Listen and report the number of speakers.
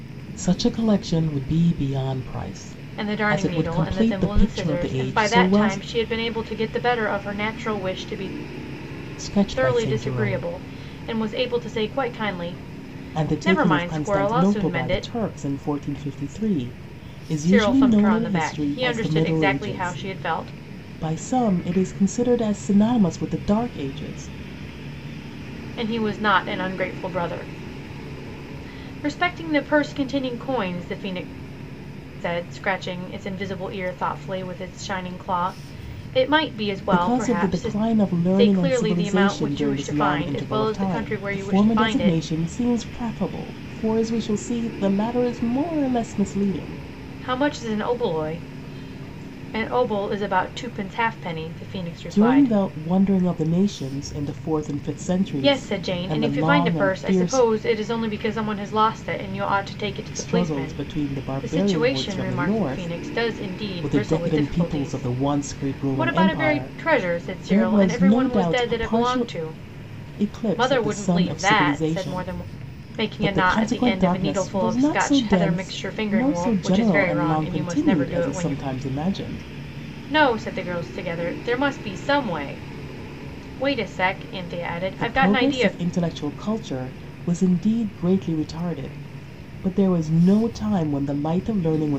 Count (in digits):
2